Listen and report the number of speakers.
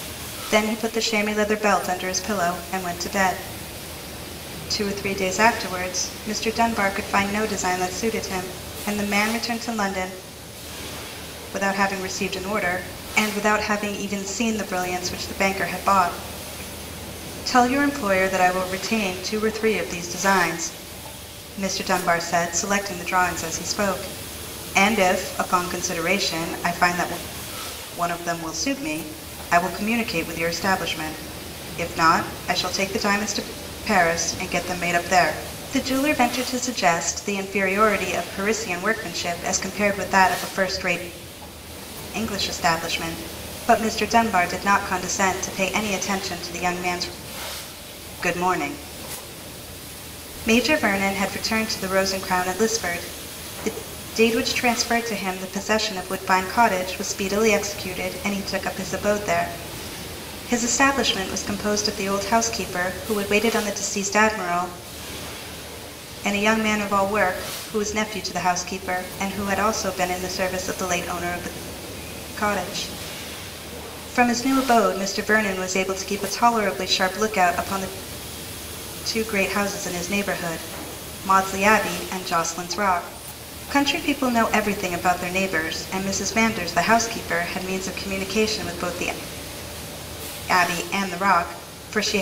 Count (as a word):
one